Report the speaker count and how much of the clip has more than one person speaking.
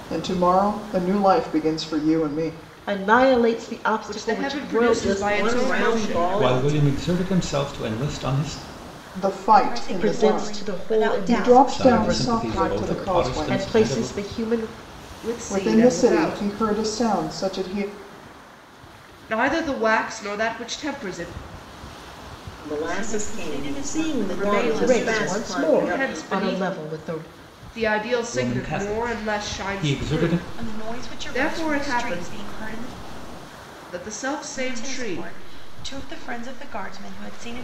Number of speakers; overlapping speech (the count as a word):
six, about 46%